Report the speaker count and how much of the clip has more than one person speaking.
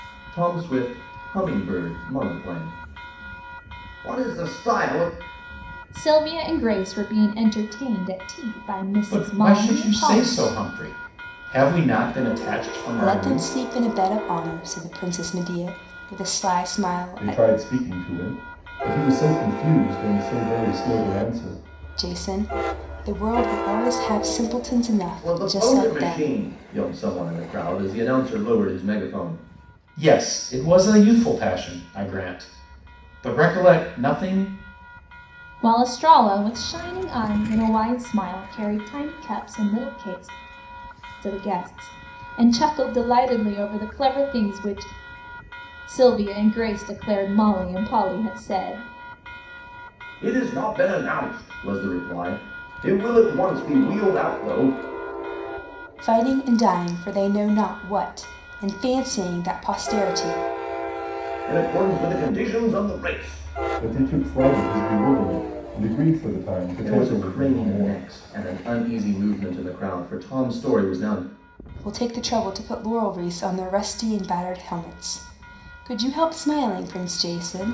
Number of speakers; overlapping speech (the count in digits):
5, about 6%